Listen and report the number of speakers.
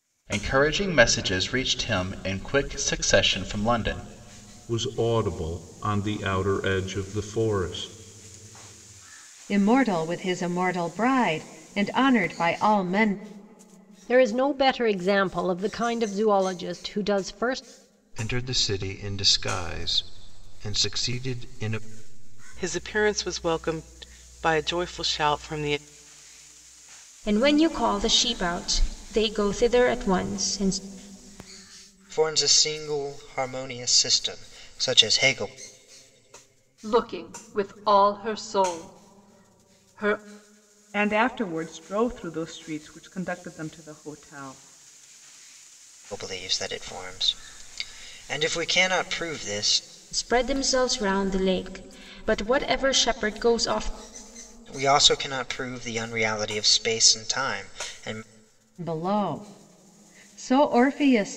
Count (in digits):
10